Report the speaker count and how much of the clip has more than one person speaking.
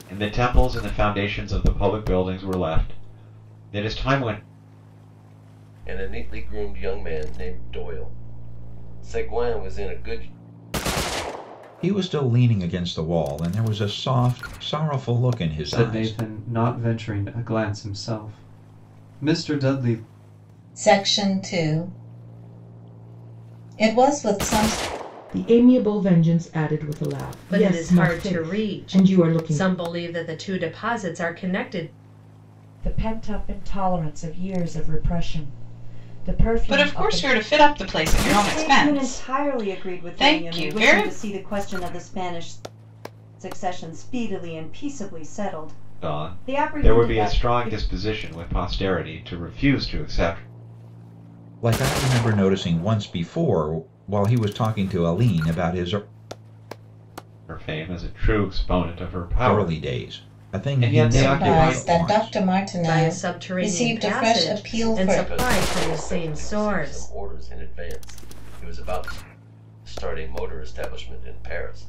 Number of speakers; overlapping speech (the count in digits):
10, about 22%